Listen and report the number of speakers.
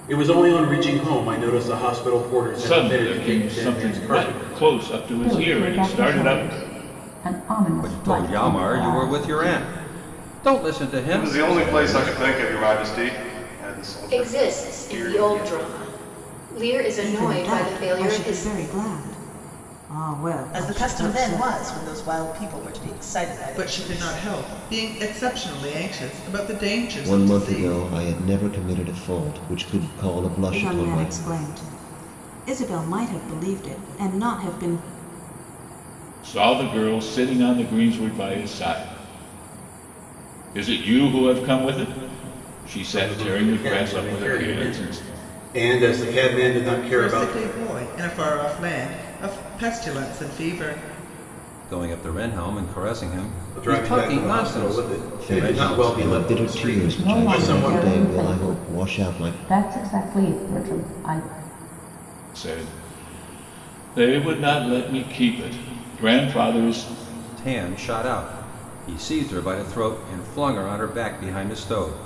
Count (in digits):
10